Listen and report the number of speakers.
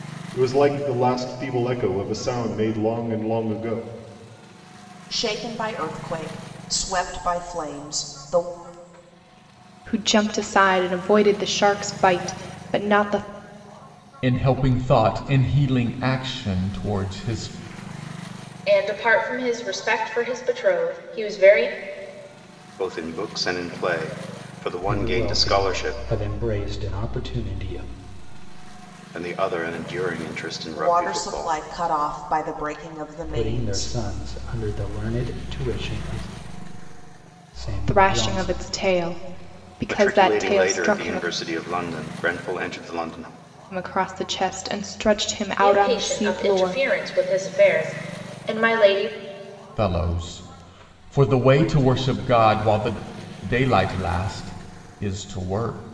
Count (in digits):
7